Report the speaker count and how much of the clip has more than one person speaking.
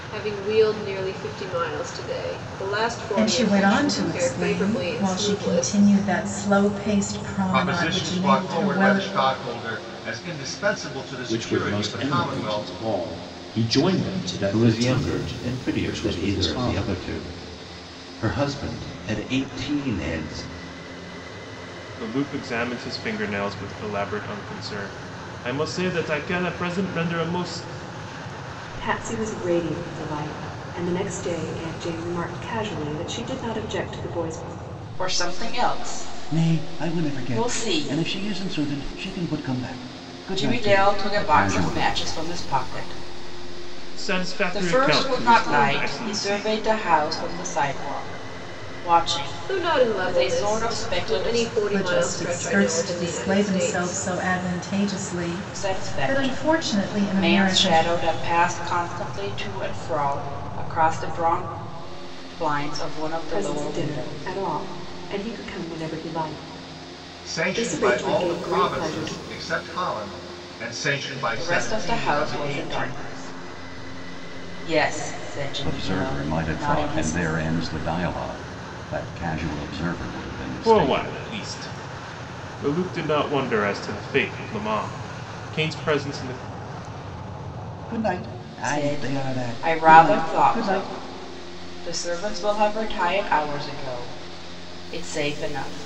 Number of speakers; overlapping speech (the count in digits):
9, about 31%